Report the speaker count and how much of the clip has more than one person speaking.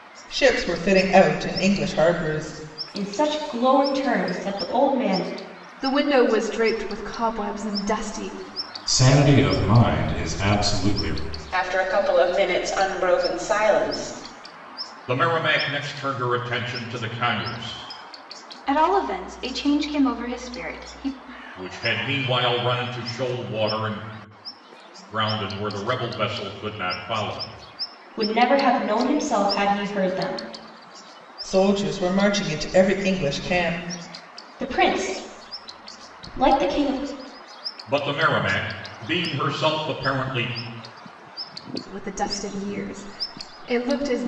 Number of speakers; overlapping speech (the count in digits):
7, no overlap